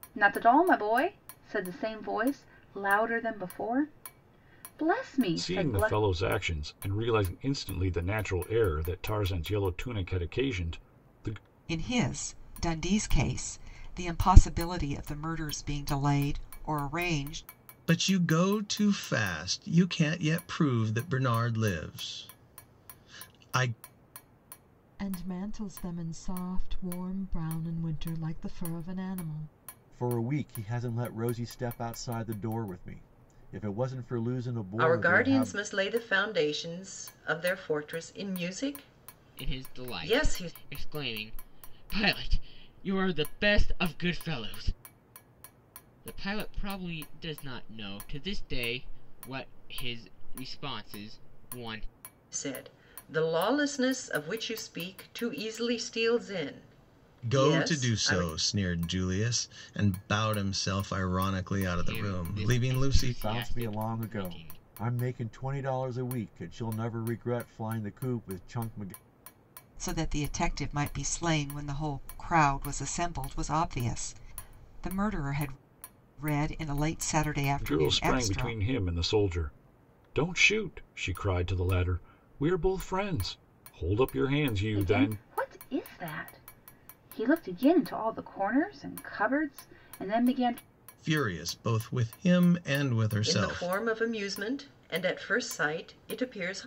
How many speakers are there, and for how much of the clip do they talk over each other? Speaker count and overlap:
8, about 9%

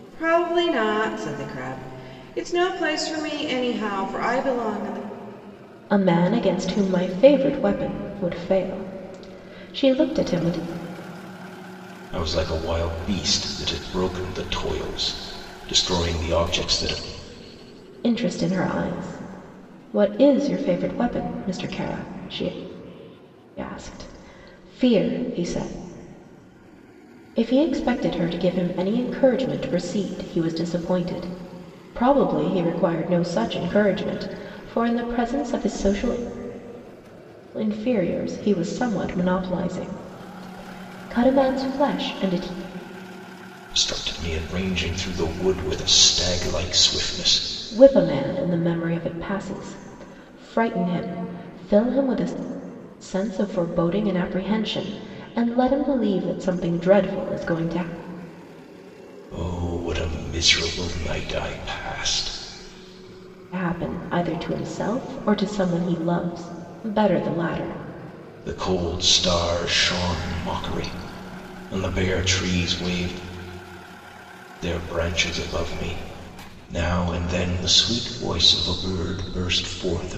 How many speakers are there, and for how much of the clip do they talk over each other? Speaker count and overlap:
3, no overlap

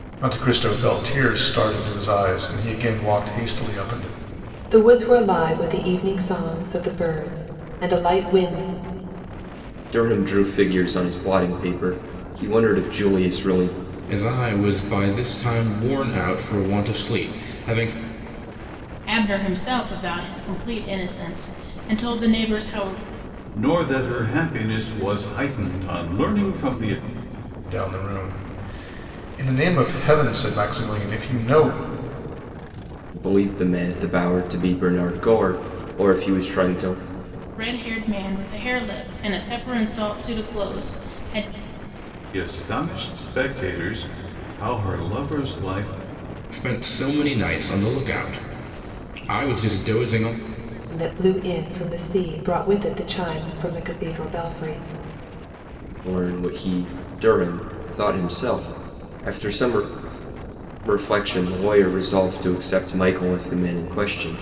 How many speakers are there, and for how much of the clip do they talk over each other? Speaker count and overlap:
6, no overlap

